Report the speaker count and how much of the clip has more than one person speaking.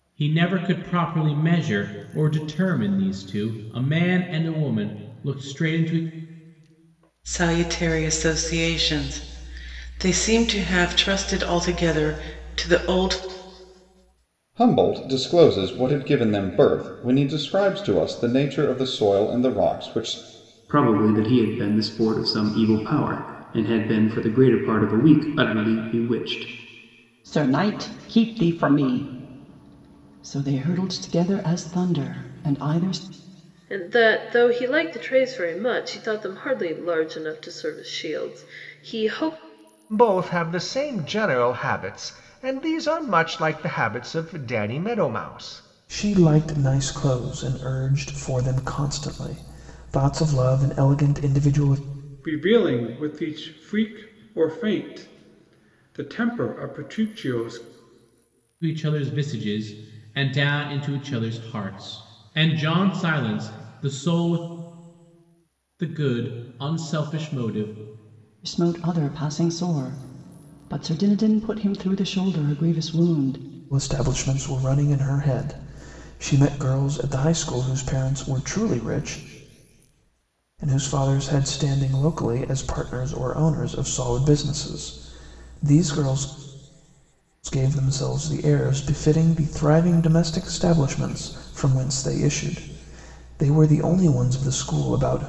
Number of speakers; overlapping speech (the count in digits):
9, no overlap